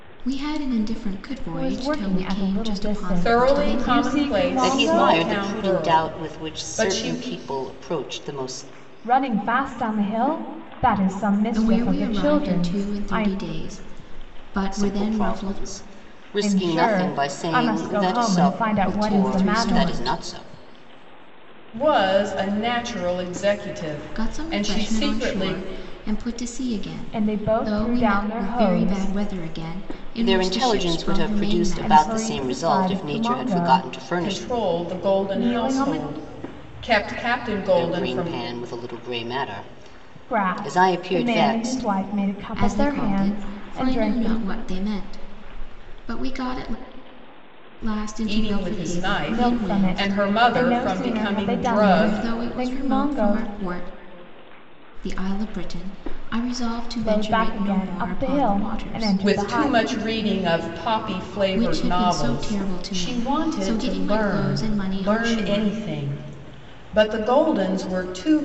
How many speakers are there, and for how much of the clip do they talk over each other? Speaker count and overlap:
4, about 55%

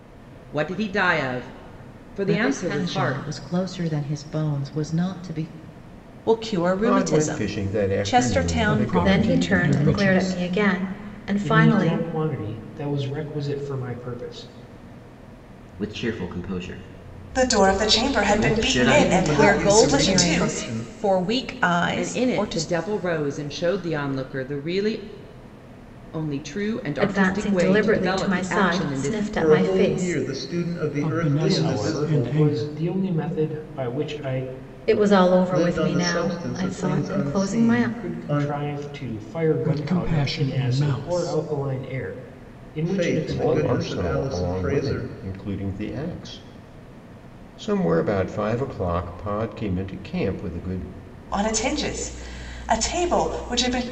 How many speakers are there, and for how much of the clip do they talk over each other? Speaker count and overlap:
10, about 41%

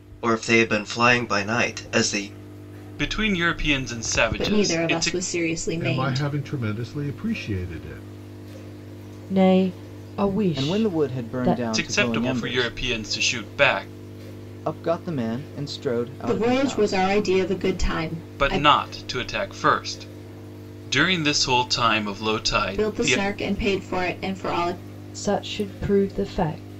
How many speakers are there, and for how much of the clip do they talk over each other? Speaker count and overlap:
6, about 20%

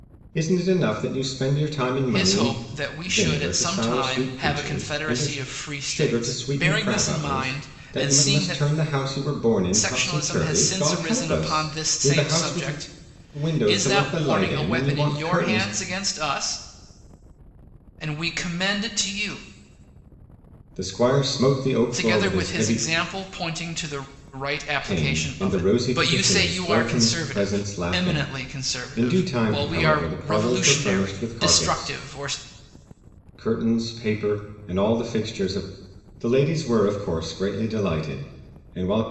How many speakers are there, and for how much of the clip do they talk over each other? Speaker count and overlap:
2, about 48%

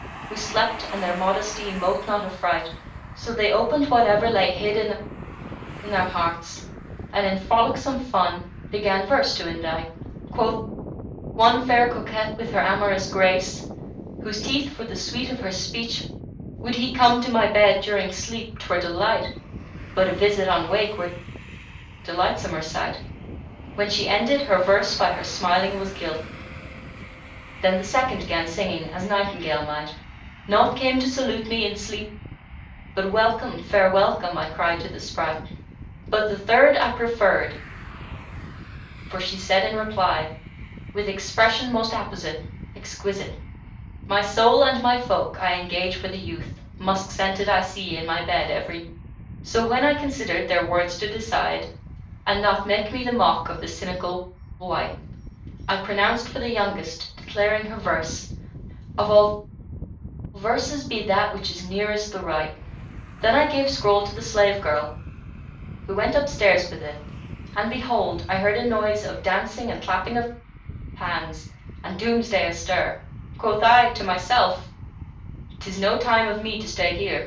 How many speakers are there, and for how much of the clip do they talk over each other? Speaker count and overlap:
1, no overlap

